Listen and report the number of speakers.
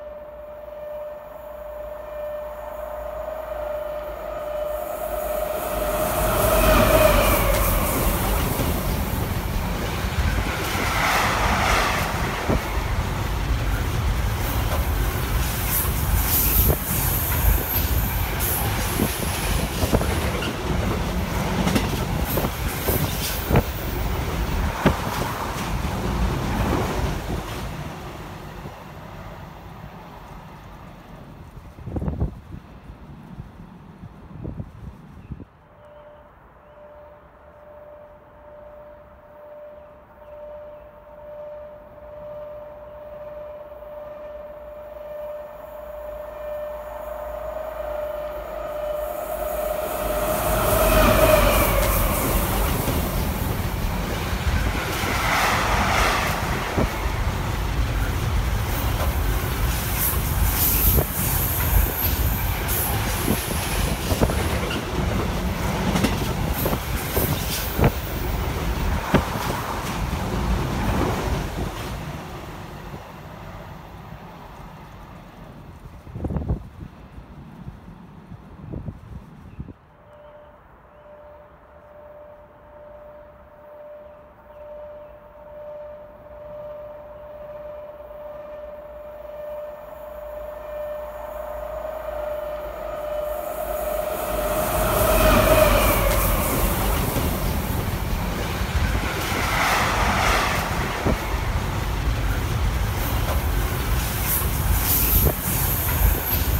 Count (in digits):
0